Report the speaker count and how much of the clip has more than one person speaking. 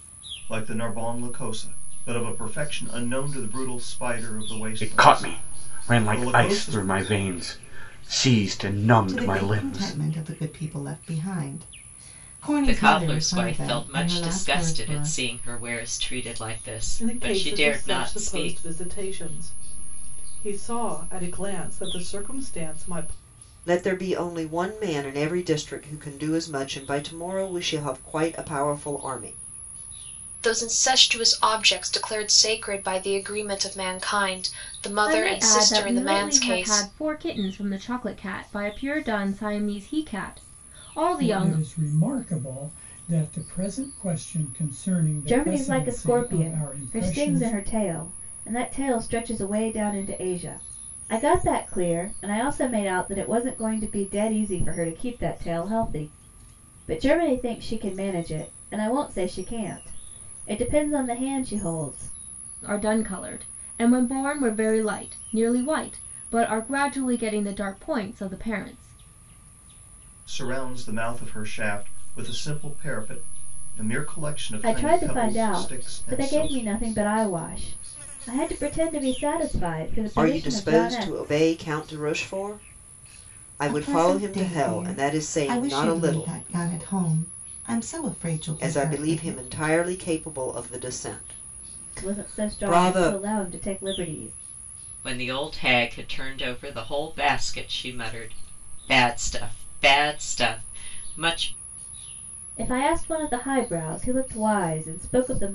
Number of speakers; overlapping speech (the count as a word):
ten, about 19%